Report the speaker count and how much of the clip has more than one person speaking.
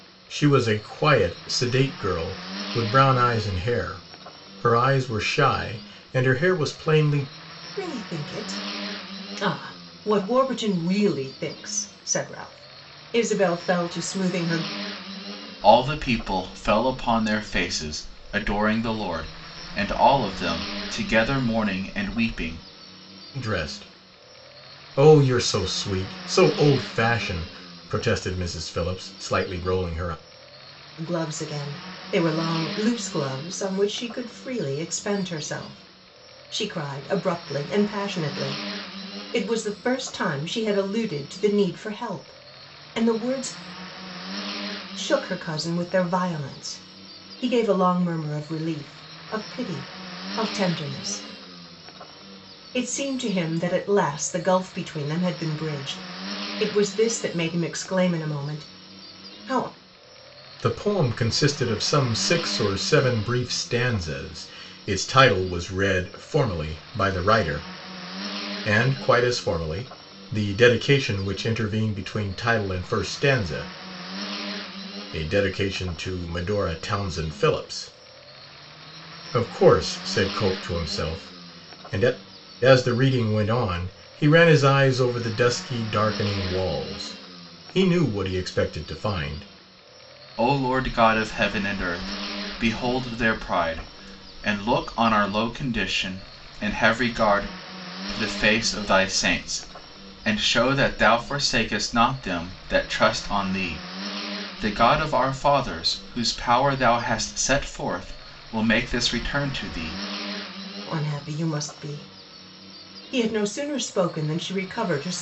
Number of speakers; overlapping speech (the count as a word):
three, no overlap